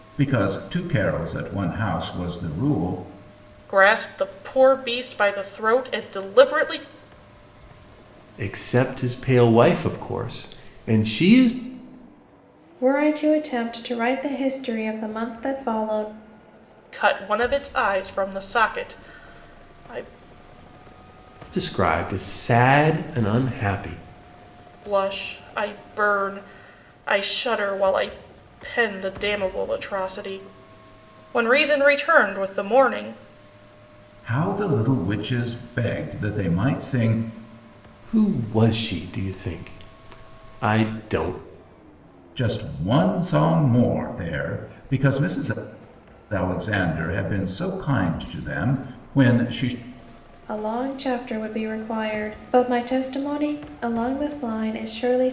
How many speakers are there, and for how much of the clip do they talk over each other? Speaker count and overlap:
four, no overlap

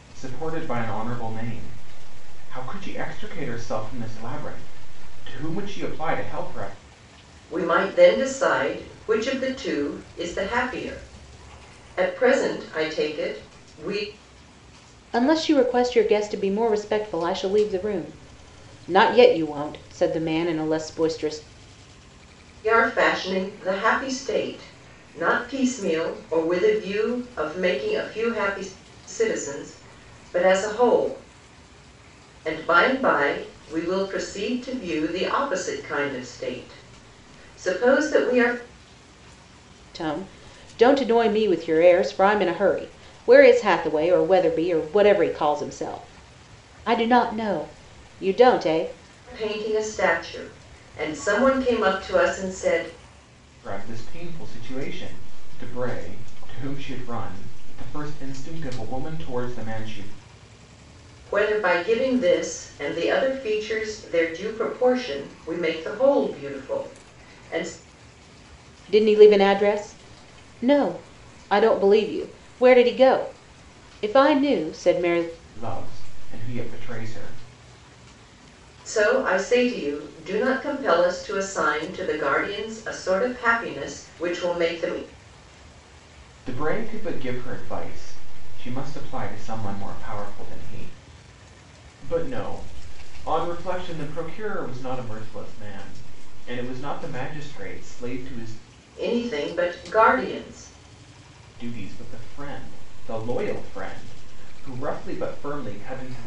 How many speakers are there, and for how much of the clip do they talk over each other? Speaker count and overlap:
three, no overlap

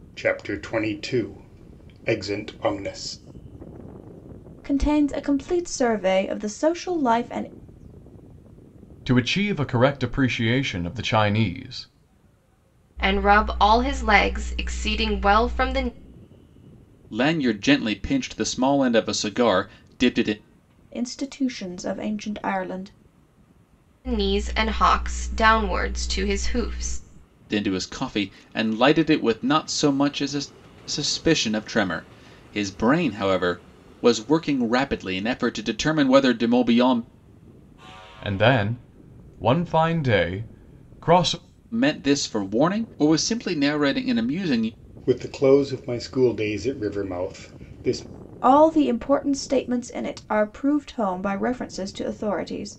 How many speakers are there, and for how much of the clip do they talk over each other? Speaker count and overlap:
five, no overlap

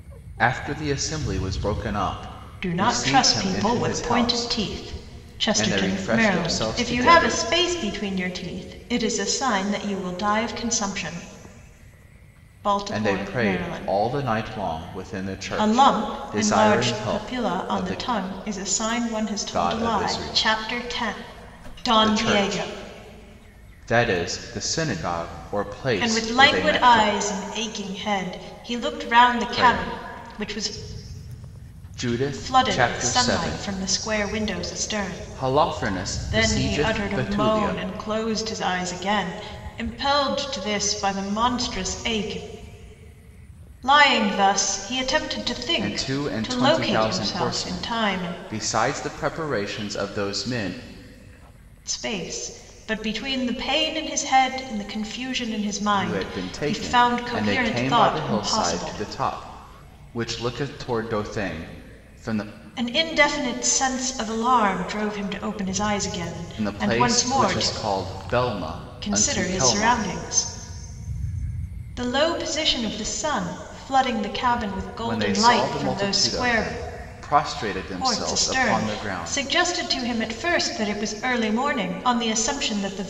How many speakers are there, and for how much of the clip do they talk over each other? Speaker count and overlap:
two, about 32%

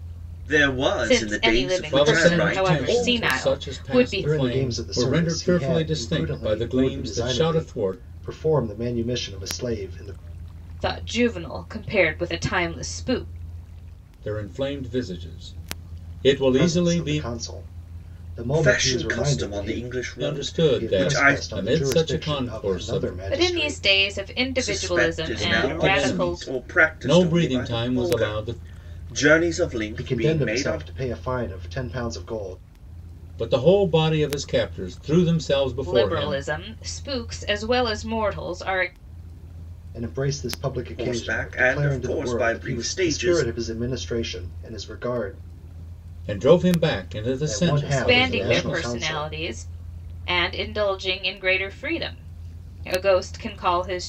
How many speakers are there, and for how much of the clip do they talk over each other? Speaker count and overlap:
four, about 42%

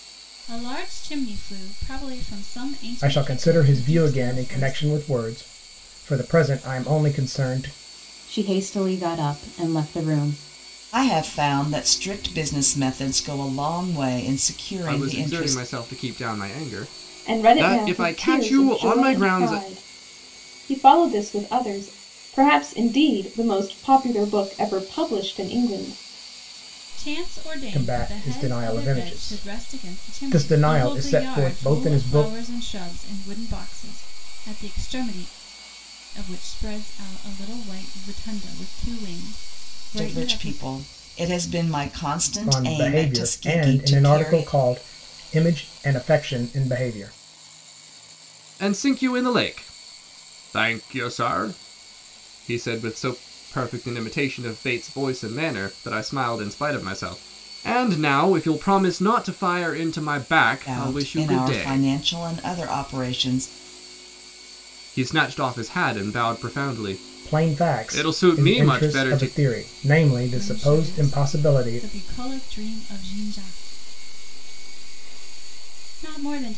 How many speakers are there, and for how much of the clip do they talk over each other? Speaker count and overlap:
six, about 23%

